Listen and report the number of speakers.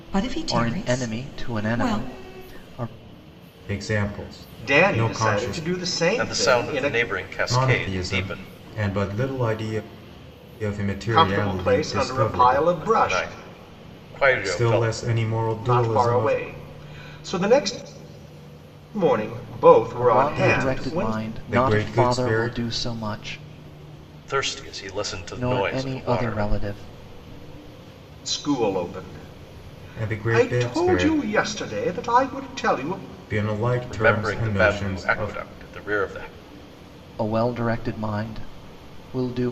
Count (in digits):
5